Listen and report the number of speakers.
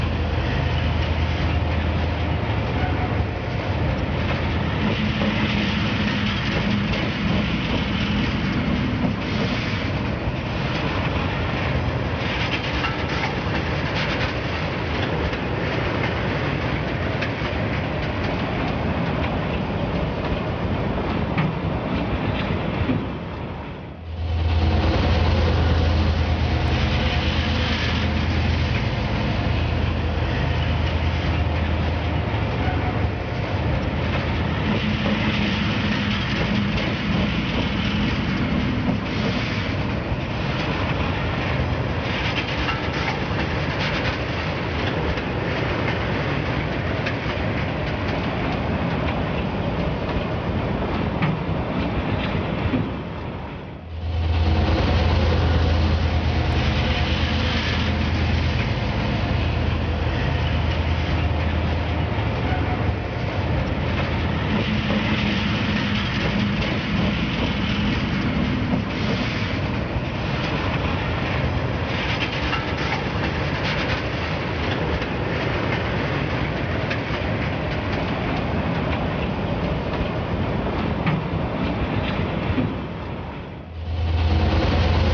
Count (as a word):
zero